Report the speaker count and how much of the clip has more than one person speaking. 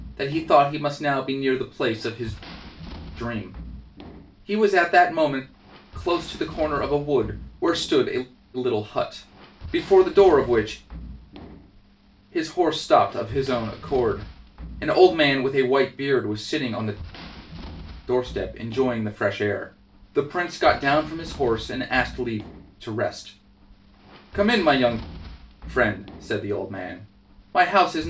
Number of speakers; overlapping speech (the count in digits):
1, no overlap